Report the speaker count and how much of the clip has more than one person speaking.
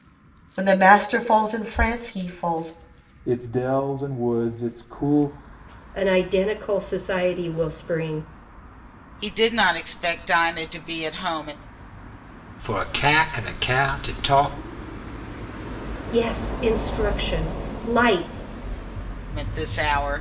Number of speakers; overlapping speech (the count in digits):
5, no overlap